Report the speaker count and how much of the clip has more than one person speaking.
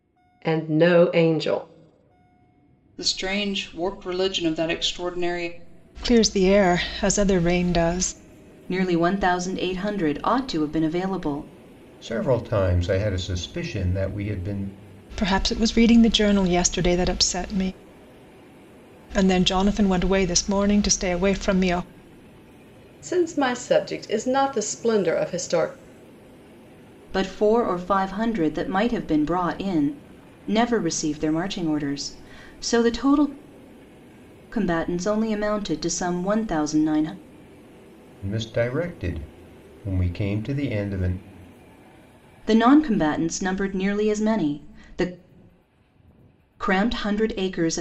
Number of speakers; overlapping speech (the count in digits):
5, no overlap